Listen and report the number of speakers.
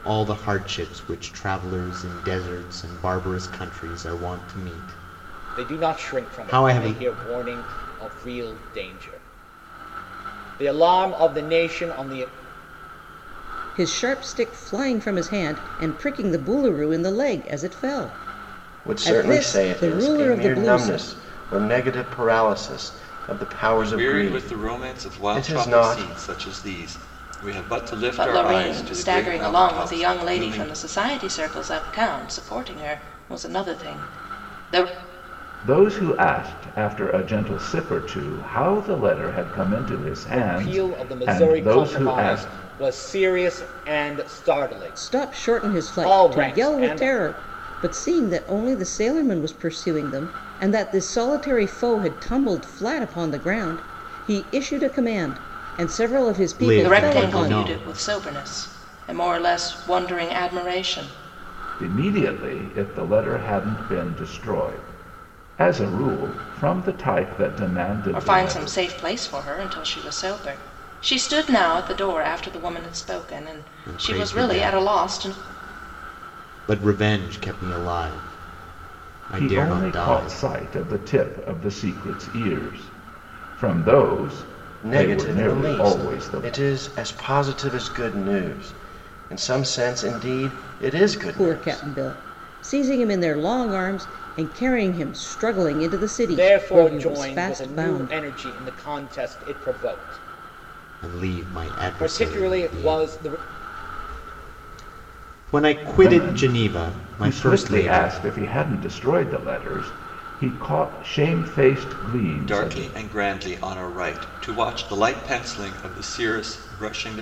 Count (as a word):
seven